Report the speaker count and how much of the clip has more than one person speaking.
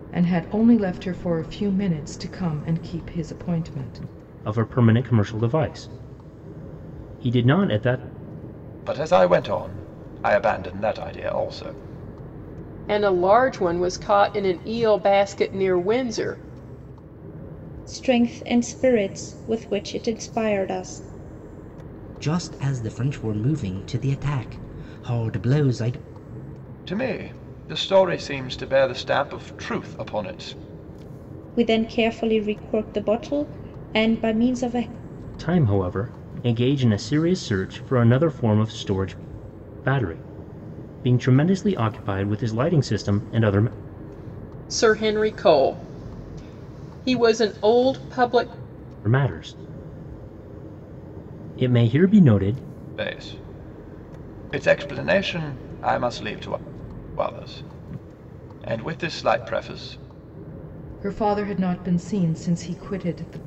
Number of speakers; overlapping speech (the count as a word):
six, no overlap